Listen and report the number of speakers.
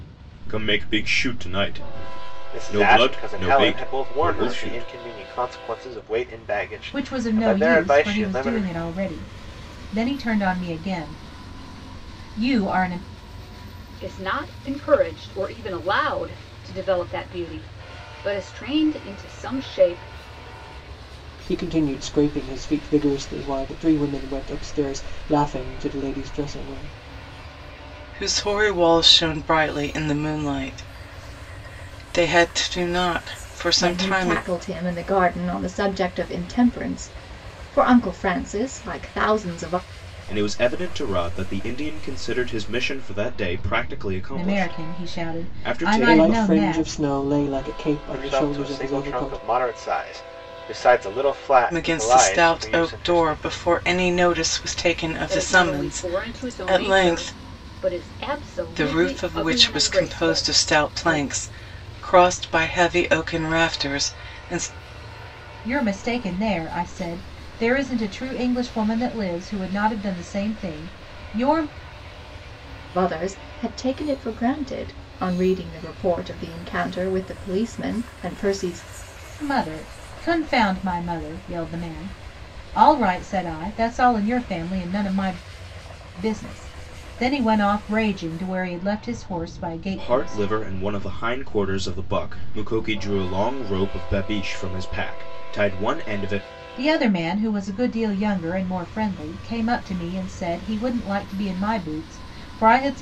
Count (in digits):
7